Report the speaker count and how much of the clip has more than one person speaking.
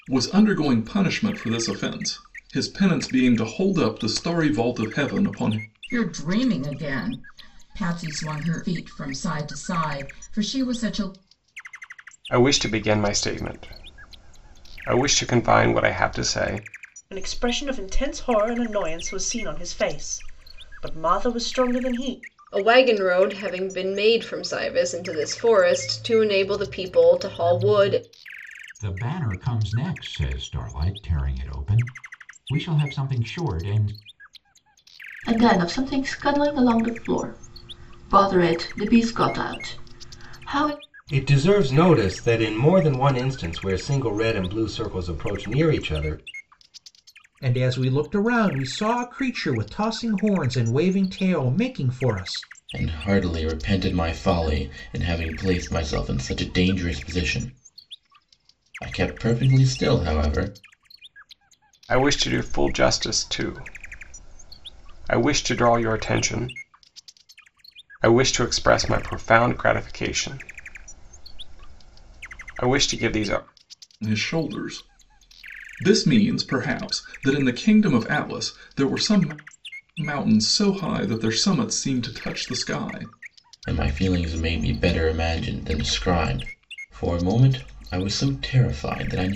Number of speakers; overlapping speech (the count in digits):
10, no overlap